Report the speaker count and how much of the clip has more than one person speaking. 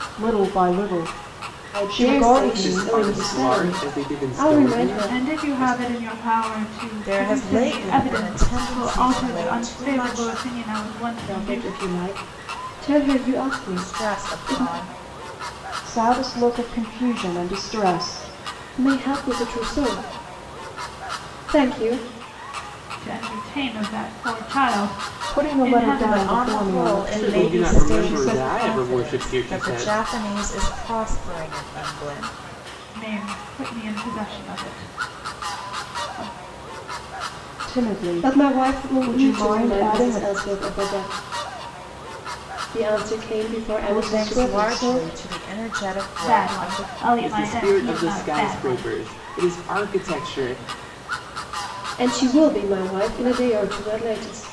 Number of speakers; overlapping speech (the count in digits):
5, about 36%